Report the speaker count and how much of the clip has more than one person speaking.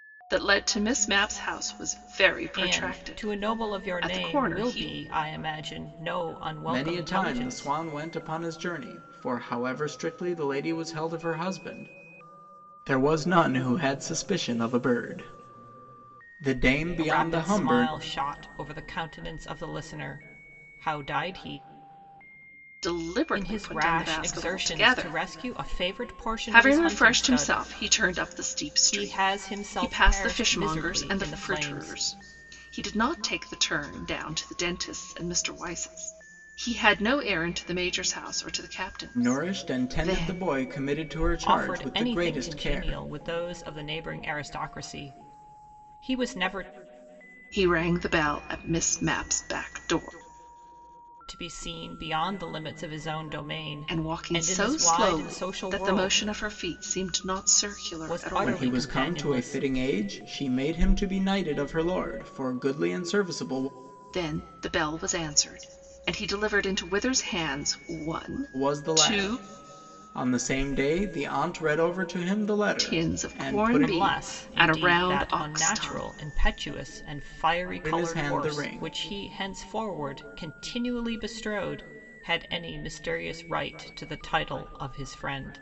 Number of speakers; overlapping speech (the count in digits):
3, about 27%